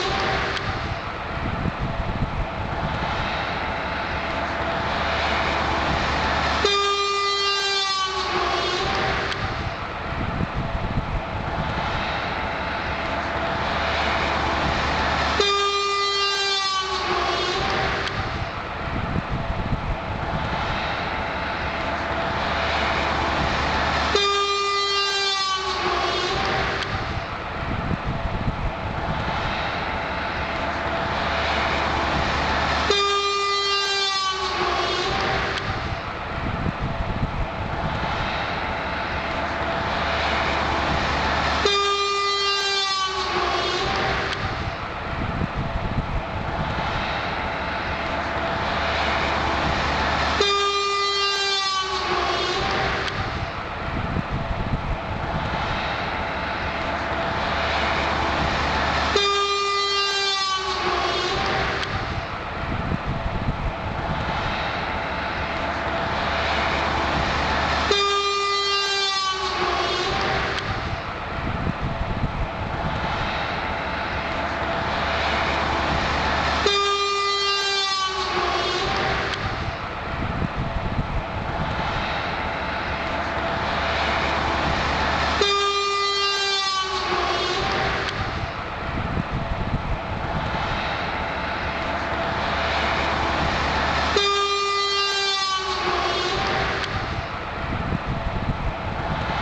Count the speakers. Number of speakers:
zero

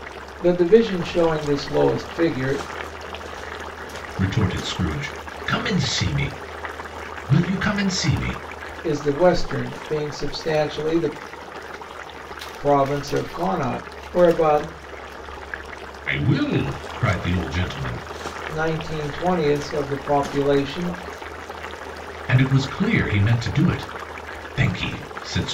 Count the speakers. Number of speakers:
two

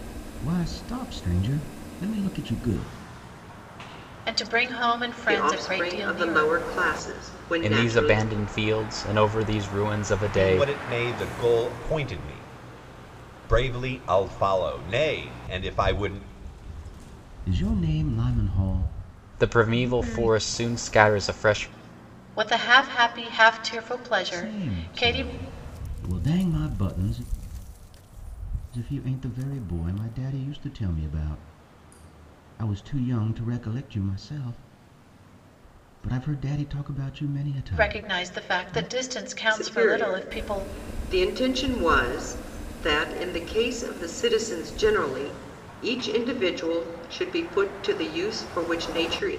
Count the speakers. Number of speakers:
five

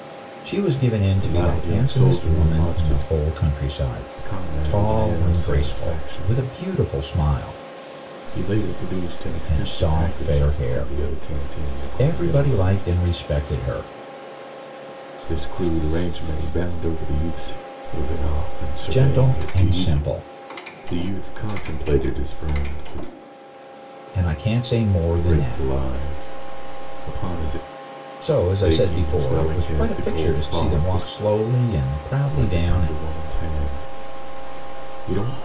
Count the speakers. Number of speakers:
two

